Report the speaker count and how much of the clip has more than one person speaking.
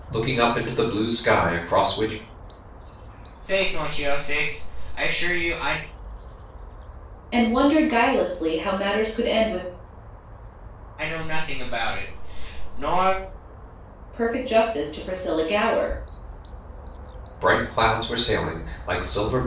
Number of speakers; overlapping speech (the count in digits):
3, no overlap